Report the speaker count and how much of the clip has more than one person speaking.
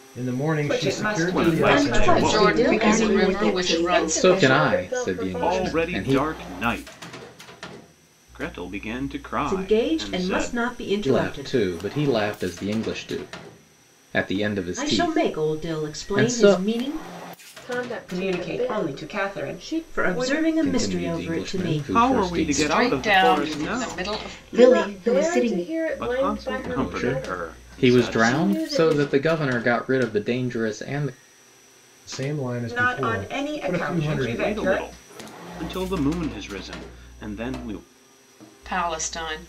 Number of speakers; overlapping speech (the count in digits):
8, about 55%